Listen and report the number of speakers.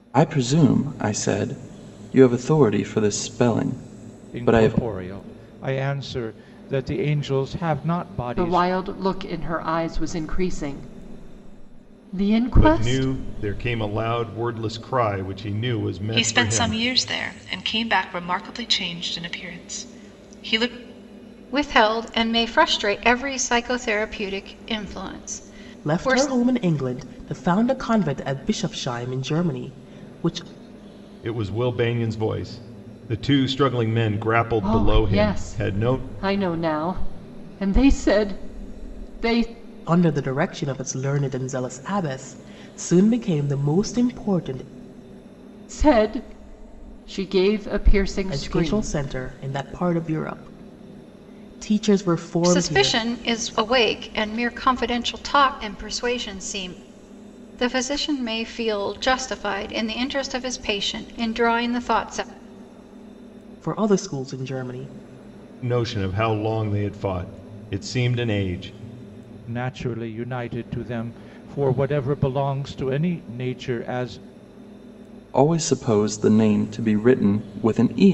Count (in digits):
7